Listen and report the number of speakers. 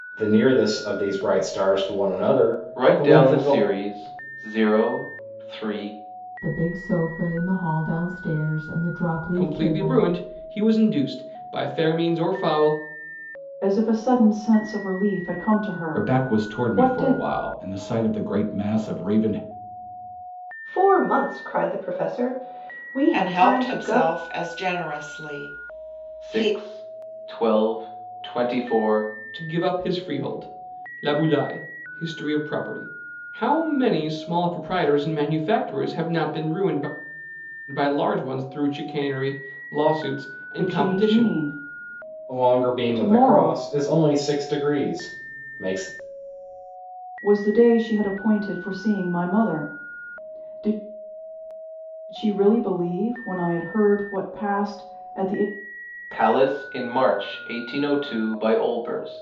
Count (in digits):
8